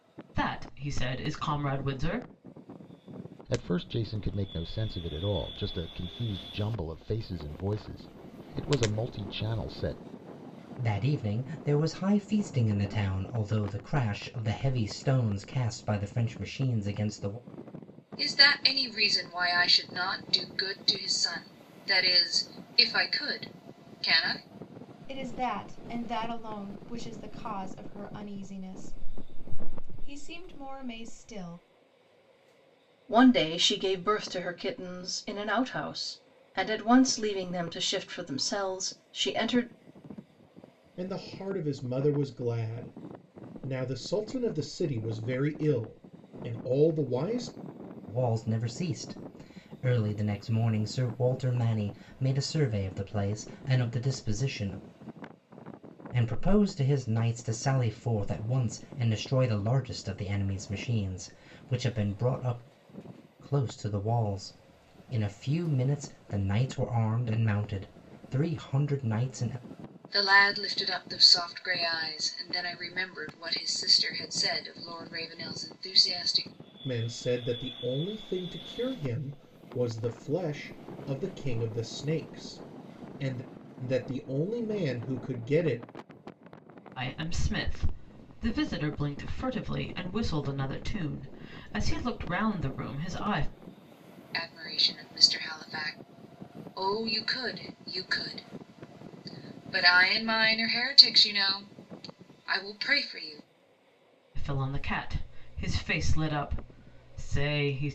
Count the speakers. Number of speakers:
7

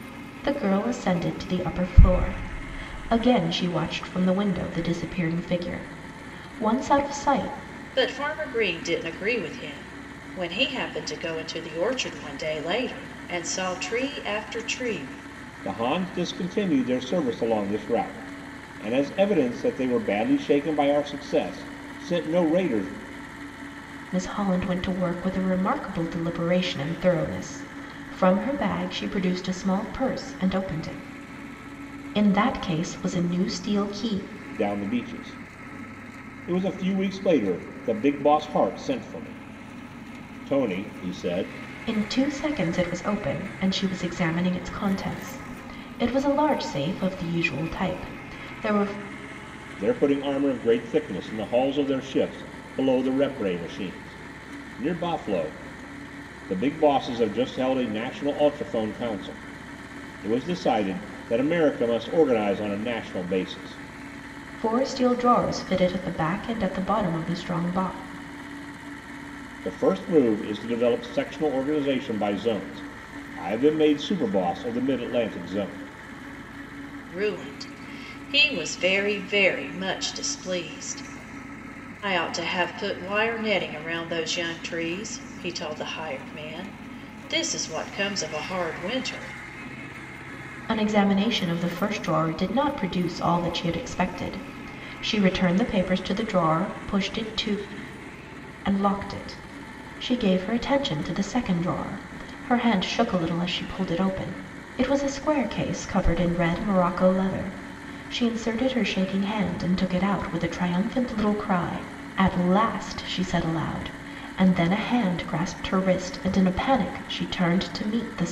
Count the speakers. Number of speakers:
3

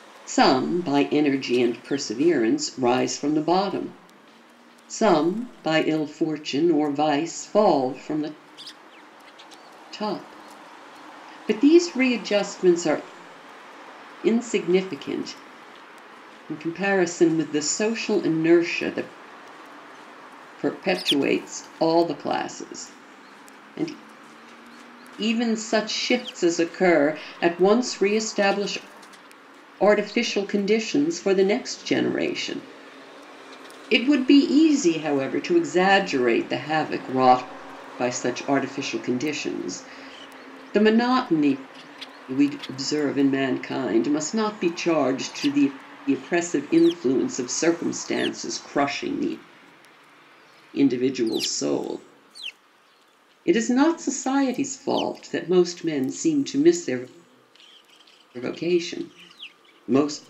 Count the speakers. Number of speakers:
1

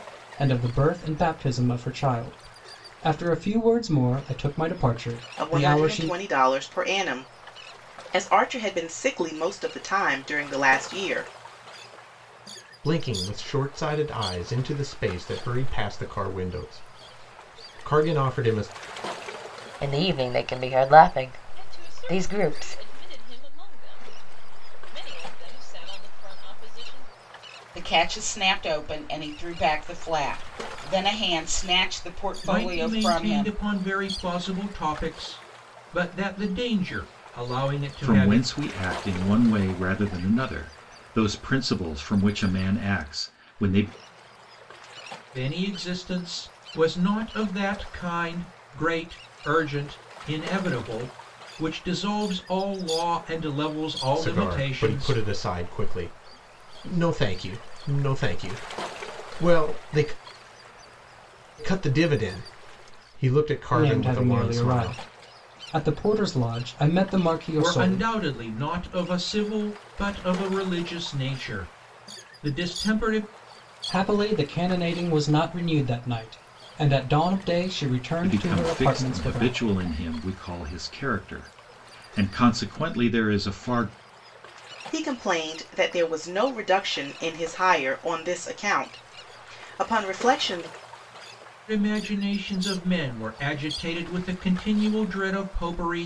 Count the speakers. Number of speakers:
8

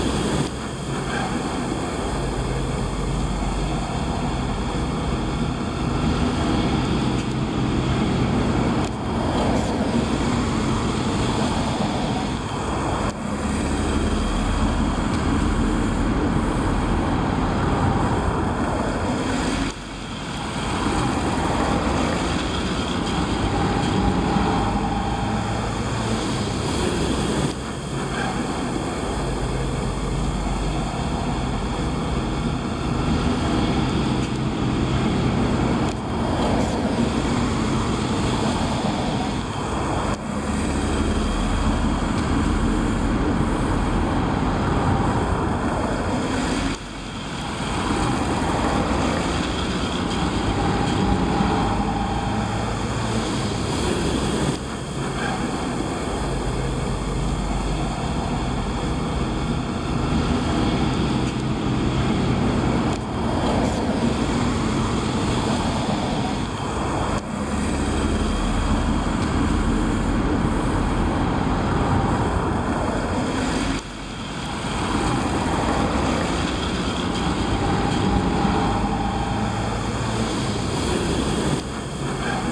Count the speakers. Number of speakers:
0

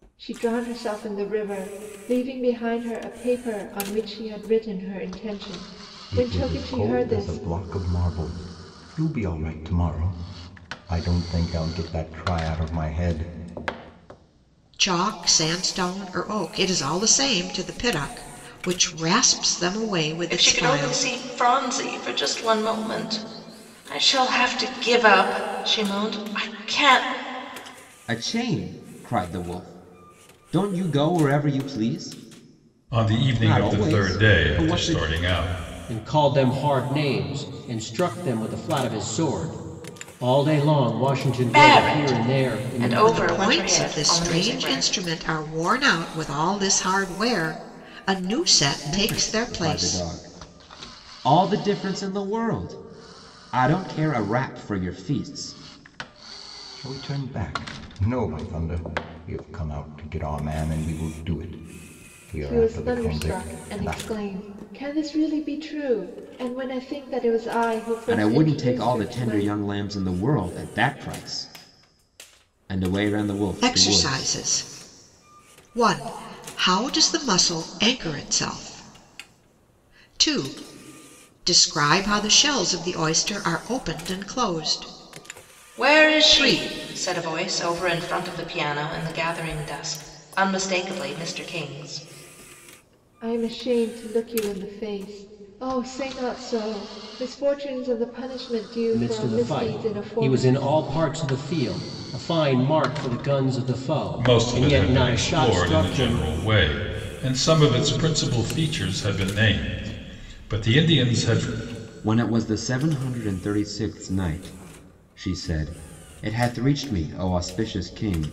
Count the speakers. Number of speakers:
7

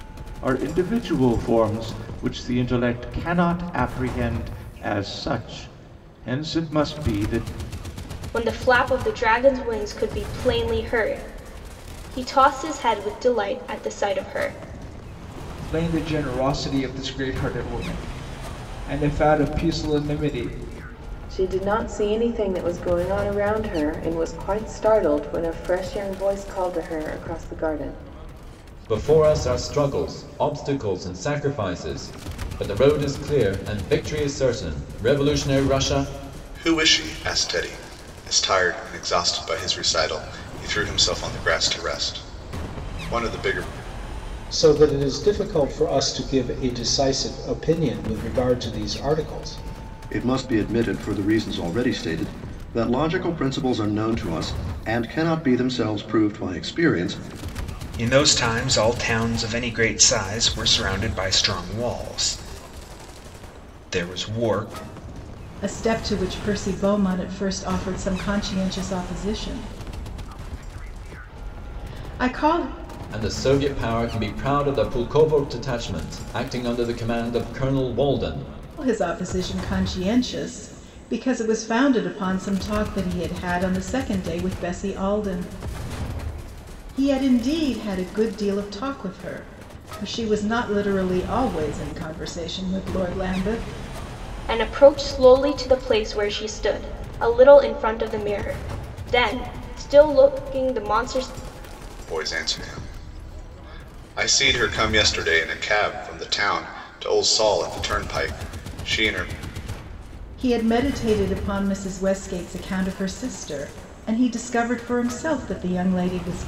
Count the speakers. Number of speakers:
10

